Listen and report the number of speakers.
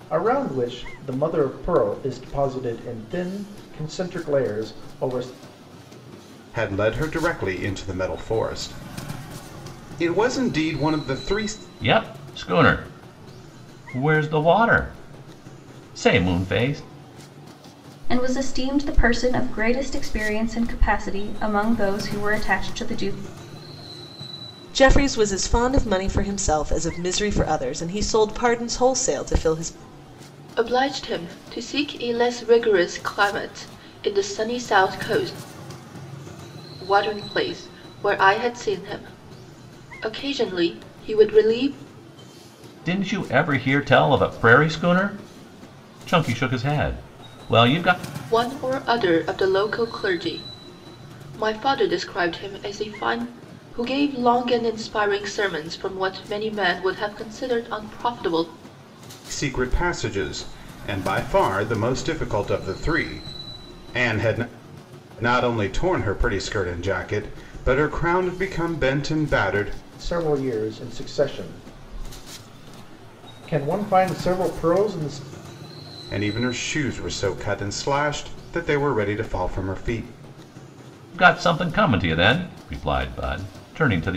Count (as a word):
six